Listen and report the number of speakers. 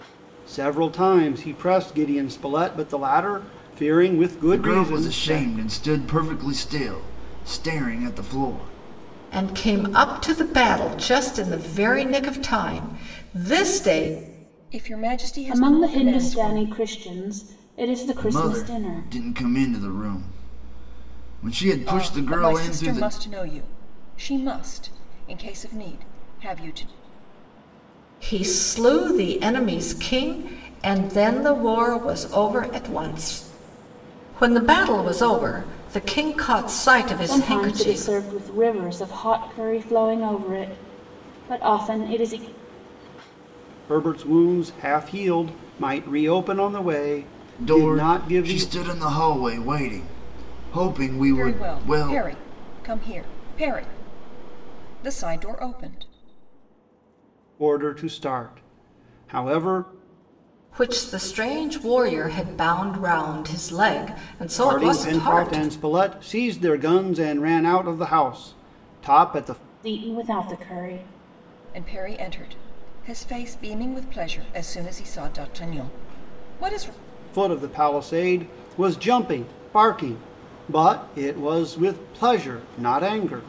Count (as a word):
five